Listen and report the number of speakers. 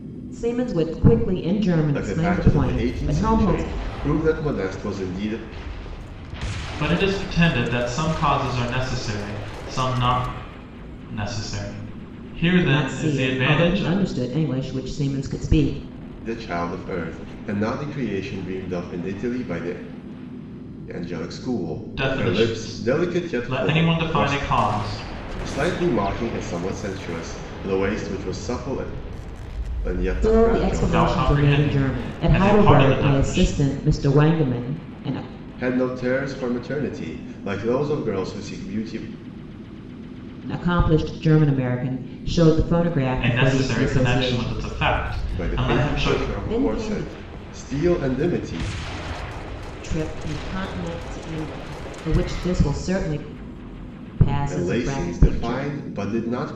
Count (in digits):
3